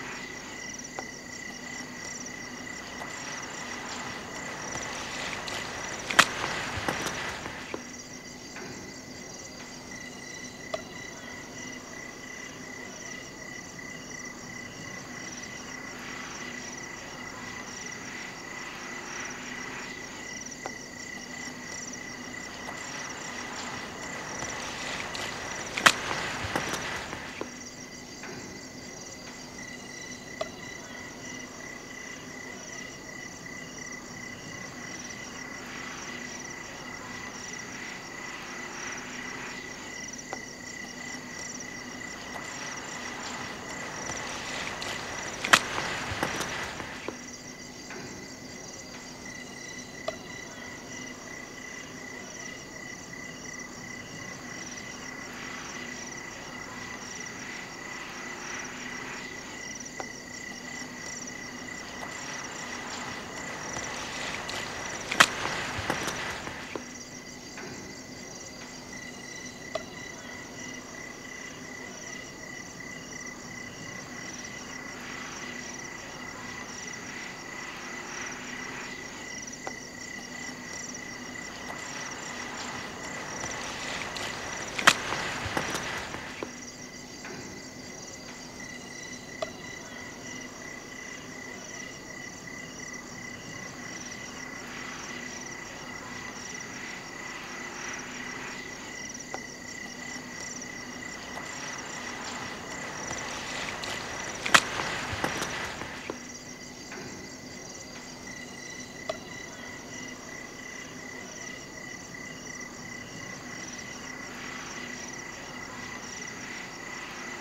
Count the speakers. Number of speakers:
0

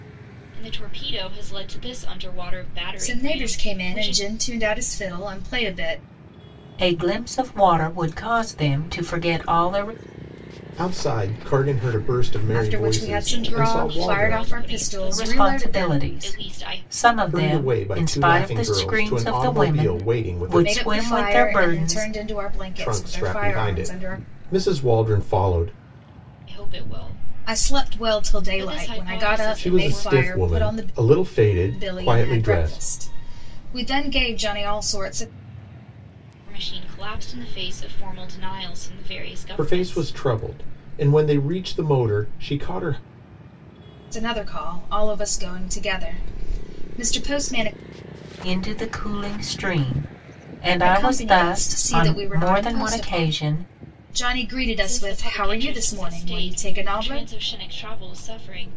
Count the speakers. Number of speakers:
4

